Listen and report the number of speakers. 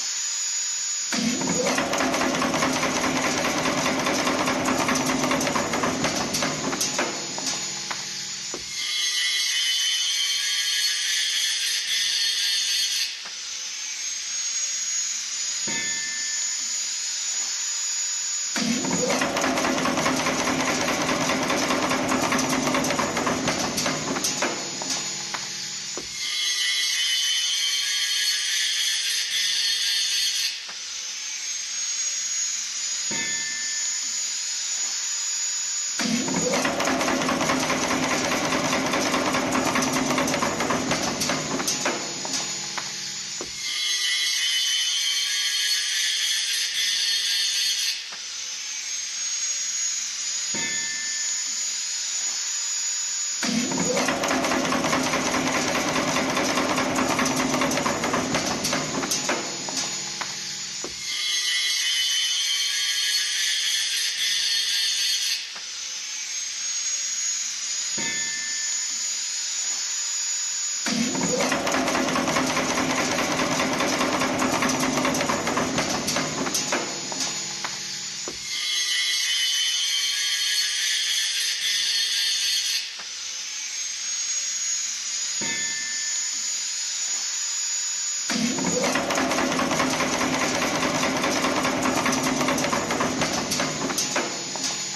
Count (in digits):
0